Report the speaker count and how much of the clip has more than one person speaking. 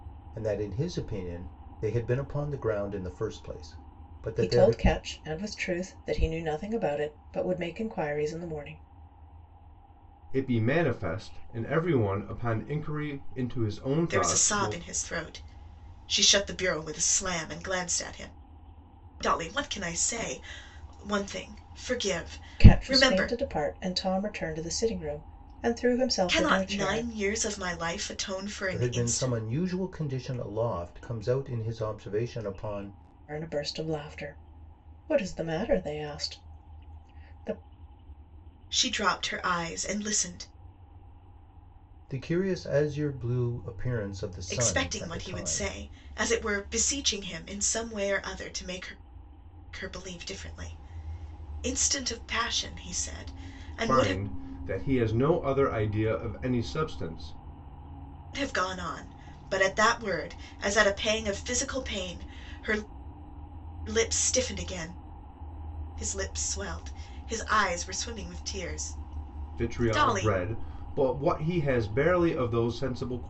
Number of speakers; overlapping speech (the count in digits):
4, about 8%